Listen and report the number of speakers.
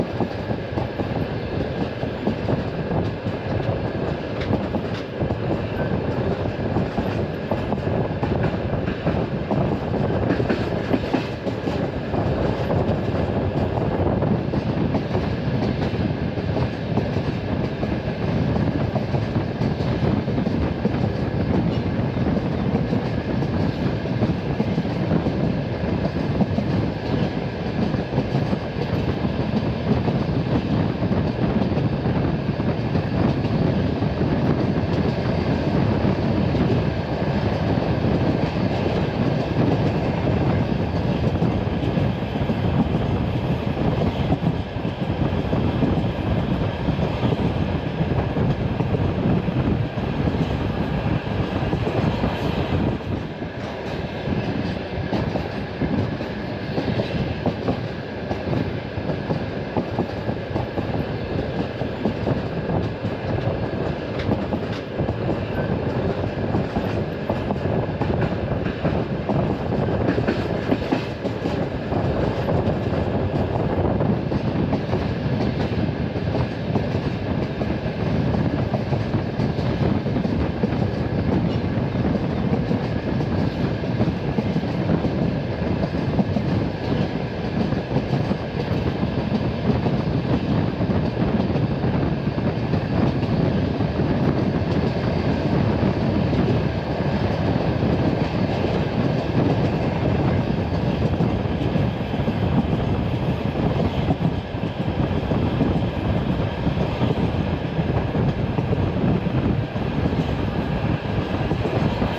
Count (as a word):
zero